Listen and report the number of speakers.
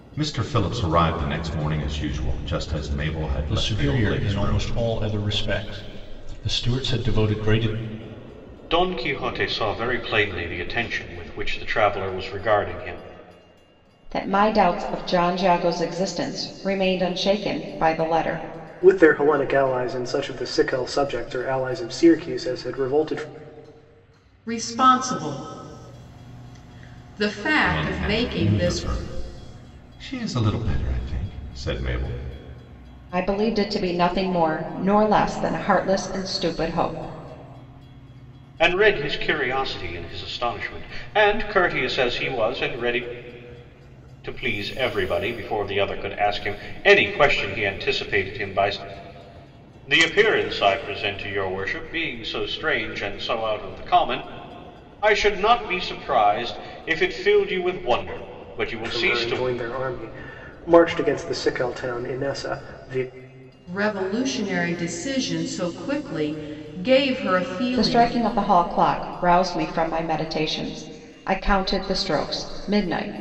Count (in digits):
6